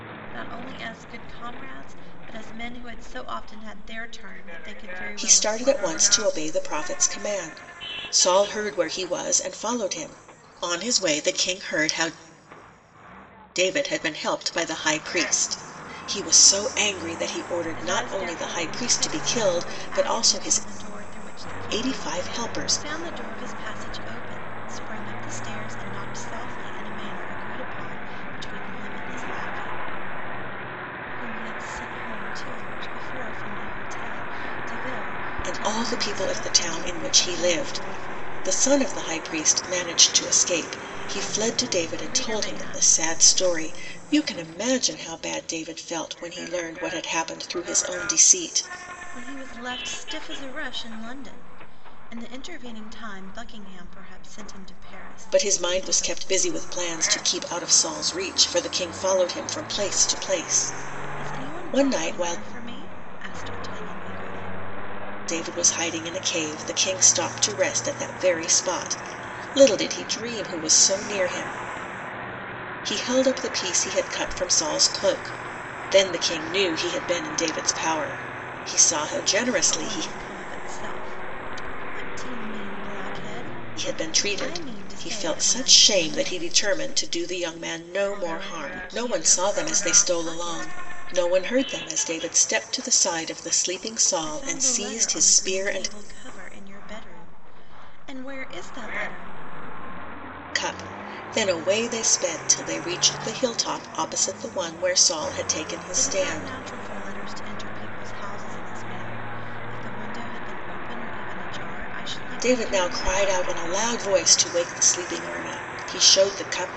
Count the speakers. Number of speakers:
2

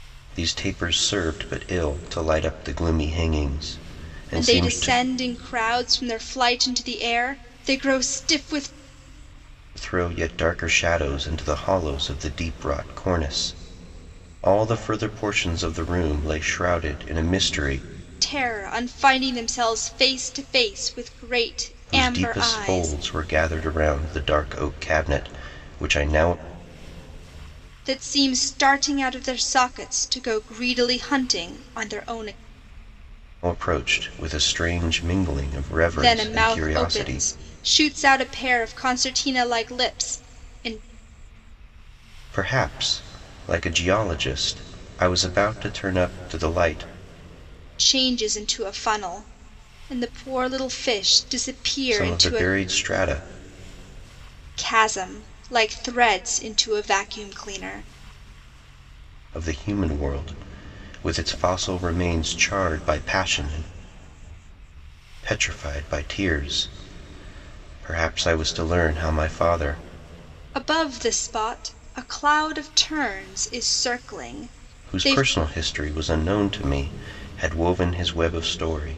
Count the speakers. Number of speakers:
2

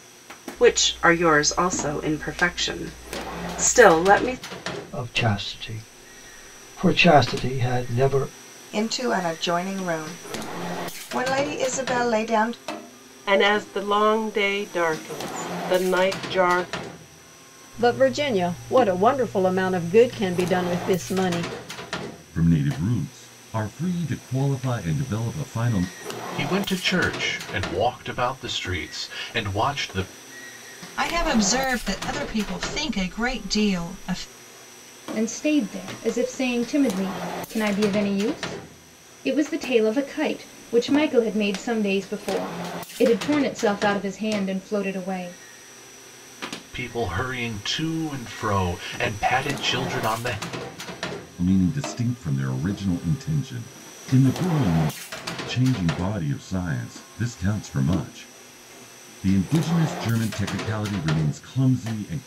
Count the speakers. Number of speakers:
9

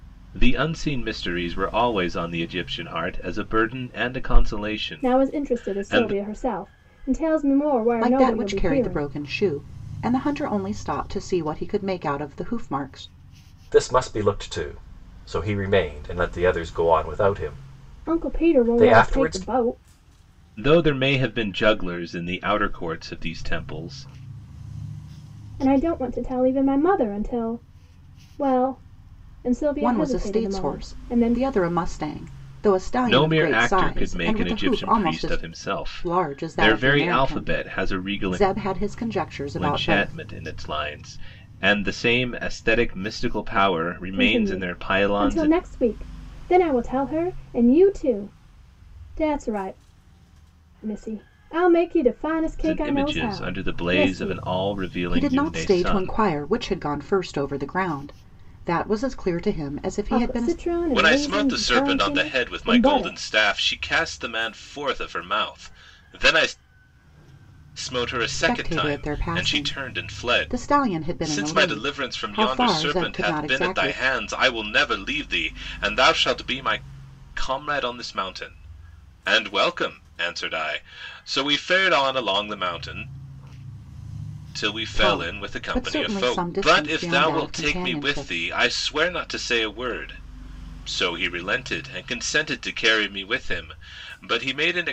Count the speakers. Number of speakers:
4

